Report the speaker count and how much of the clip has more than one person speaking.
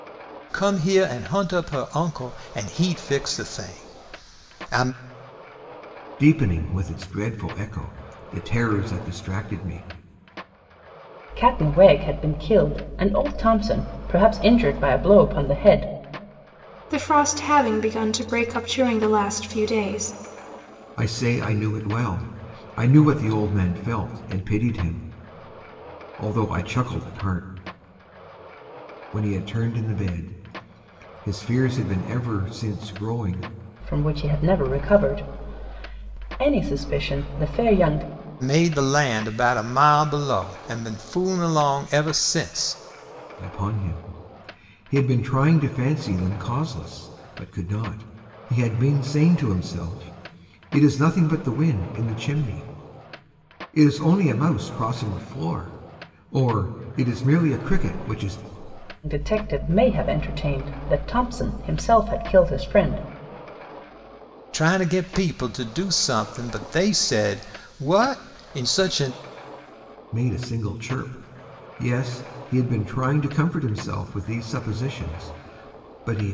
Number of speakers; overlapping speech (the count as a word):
four, no overlap